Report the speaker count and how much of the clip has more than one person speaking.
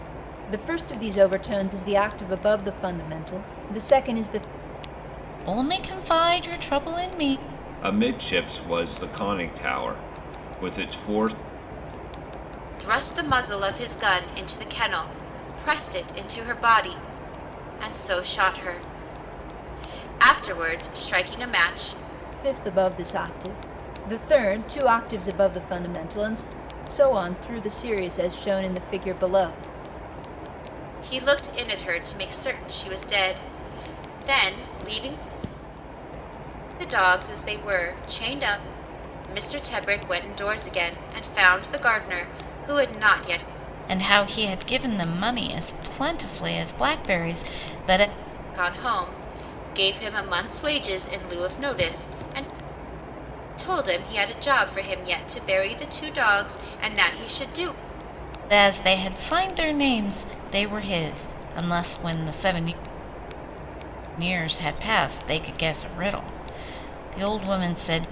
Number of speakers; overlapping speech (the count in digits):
4, no overlap